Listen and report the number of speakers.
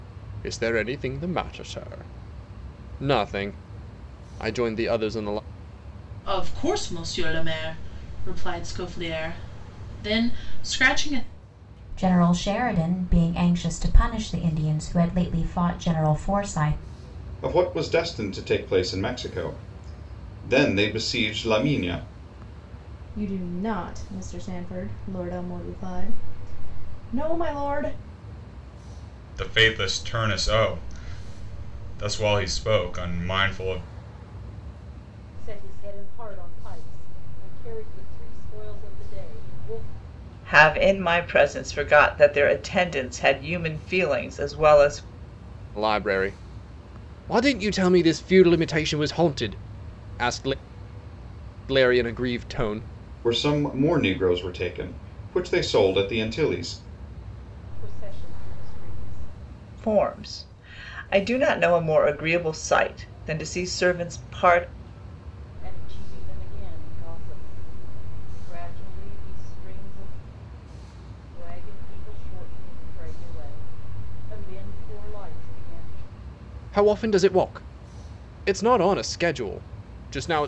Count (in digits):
8